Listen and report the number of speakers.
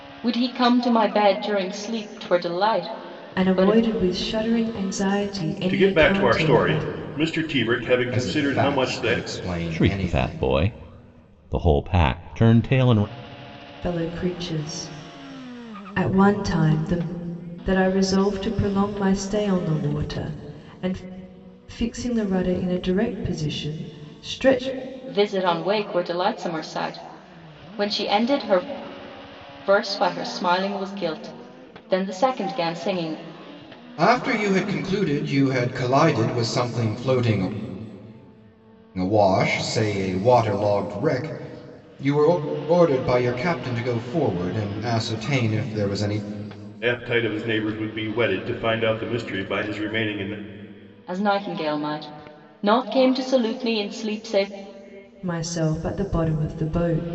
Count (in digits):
5